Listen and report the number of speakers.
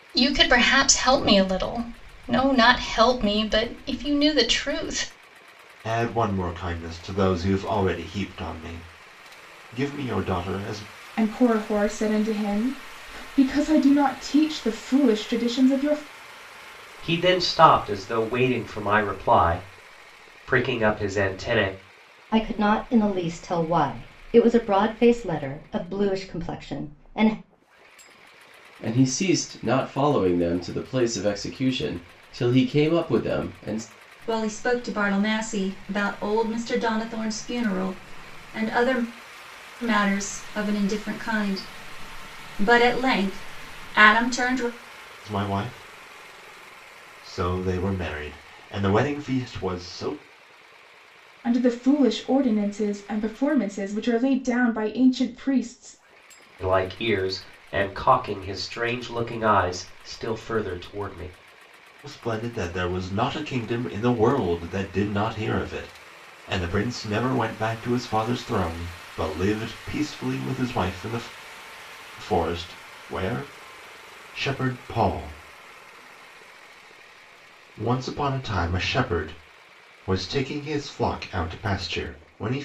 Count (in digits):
7